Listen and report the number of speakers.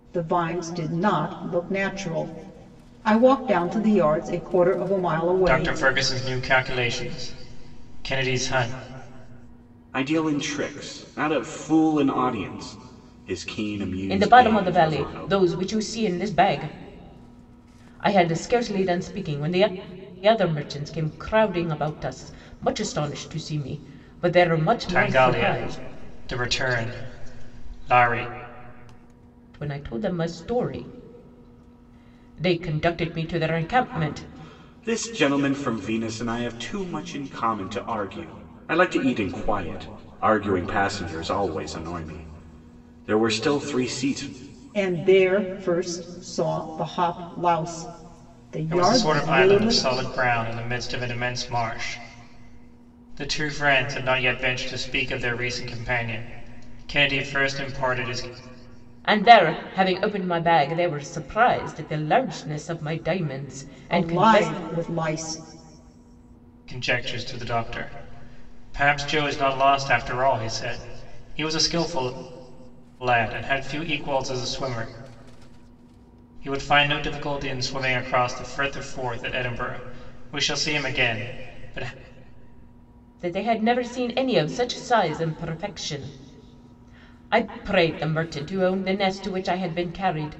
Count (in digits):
4